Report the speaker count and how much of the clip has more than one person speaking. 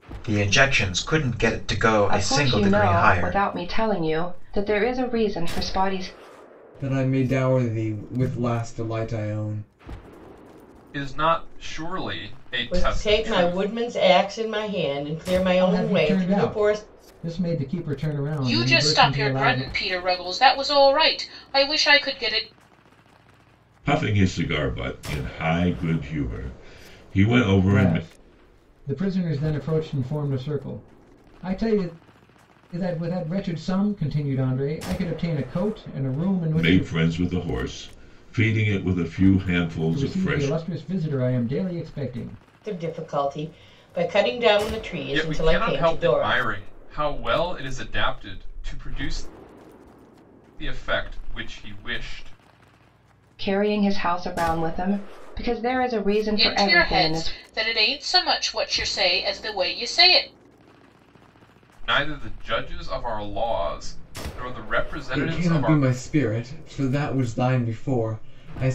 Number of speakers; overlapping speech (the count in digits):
8, about 14%